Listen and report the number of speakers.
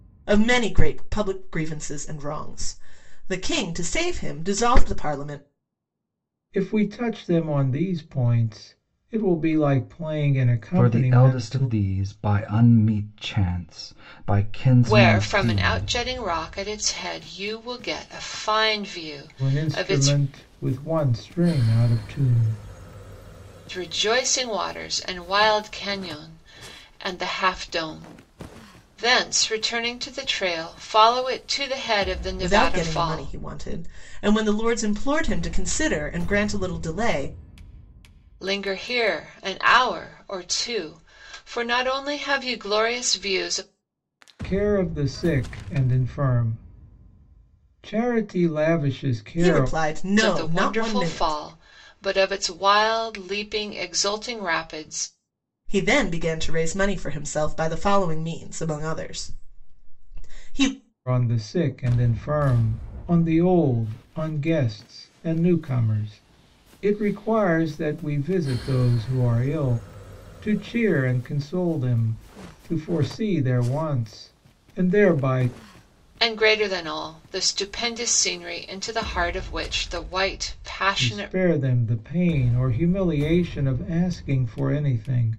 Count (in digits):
4